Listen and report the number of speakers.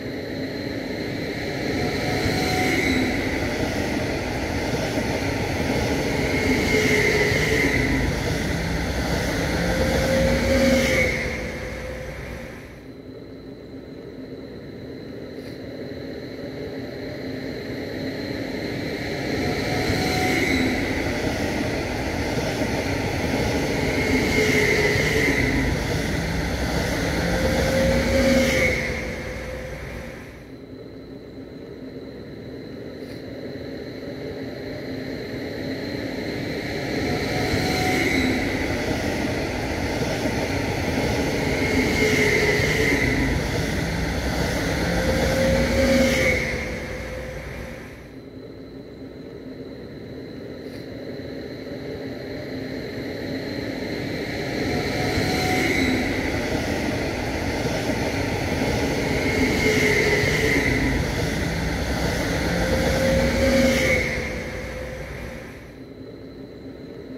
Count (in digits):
0